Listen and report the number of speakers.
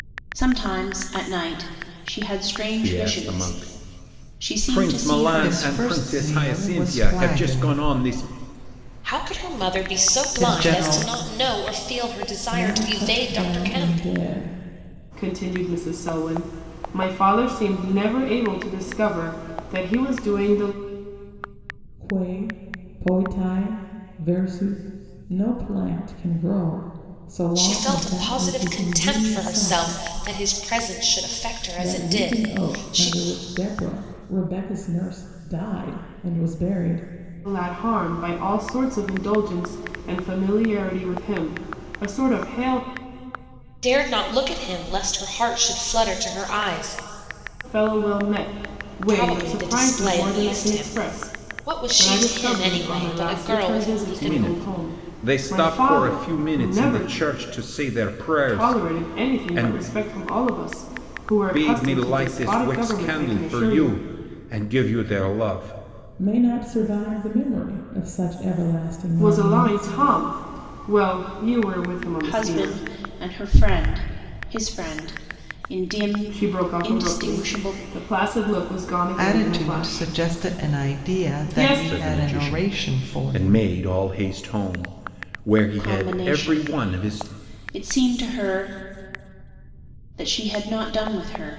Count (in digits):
6